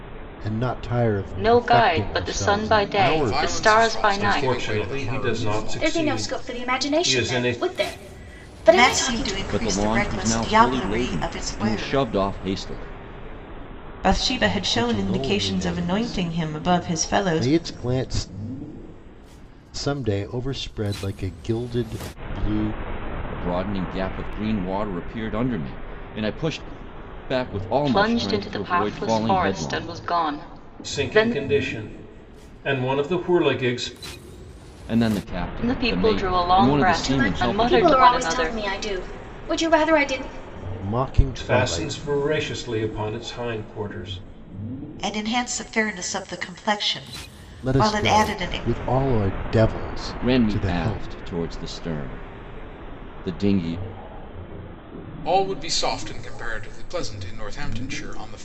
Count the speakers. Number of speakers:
8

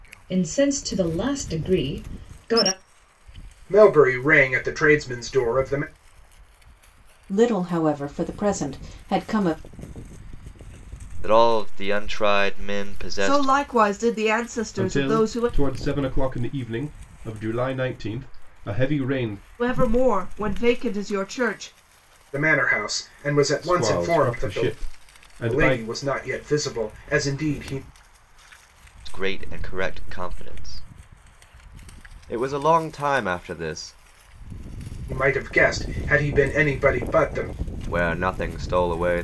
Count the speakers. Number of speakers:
6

